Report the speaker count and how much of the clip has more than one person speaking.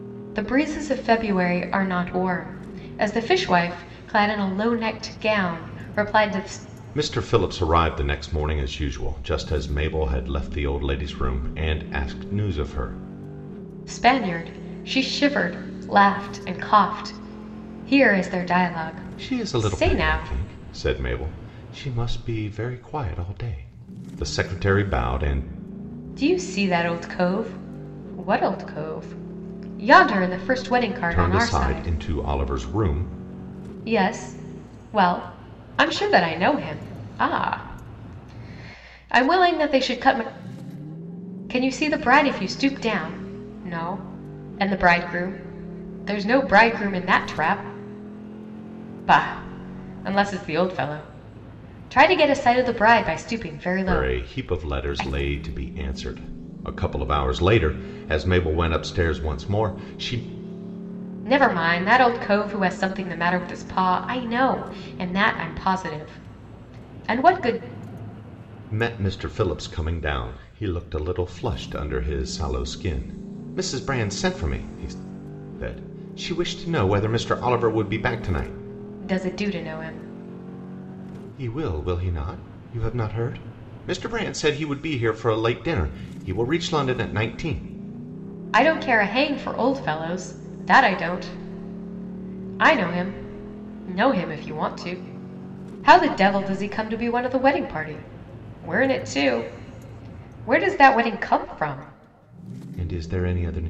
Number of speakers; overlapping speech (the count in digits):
2, about 3%